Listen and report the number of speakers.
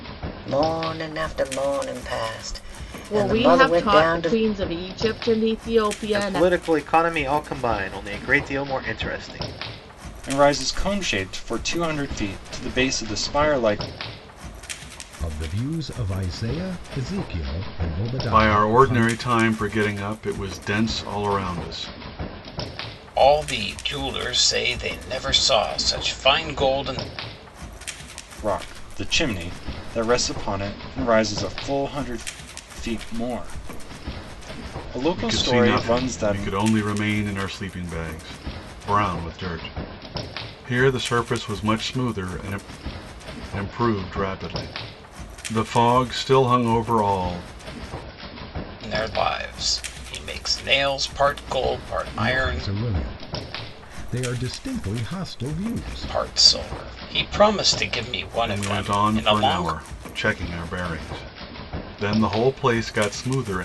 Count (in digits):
7